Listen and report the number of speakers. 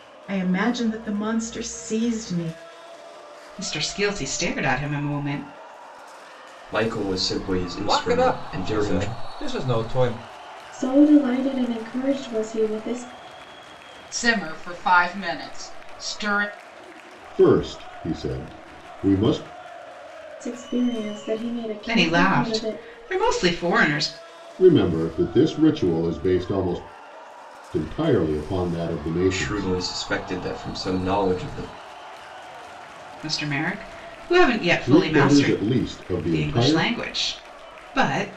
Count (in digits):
7